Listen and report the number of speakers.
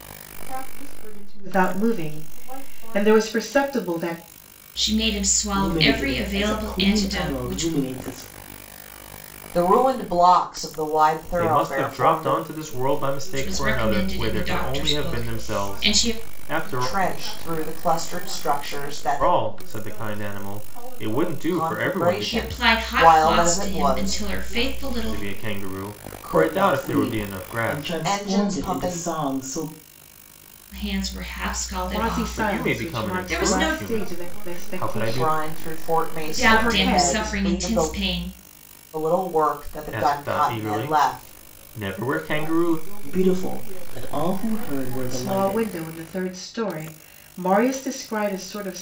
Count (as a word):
six